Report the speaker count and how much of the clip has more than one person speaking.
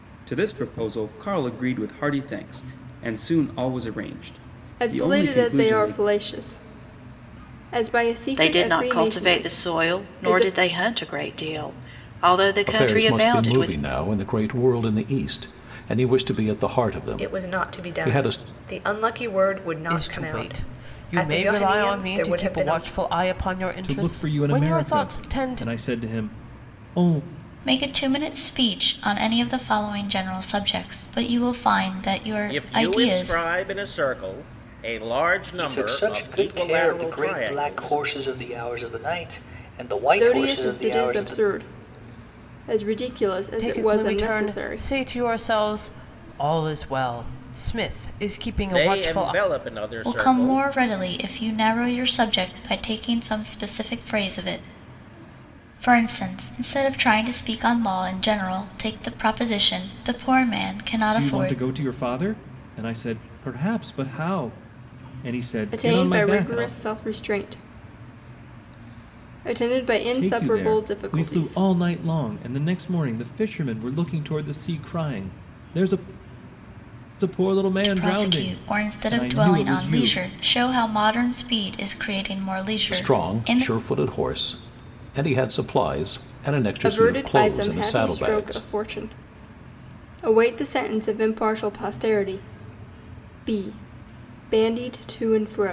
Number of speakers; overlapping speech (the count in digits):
10, about 28%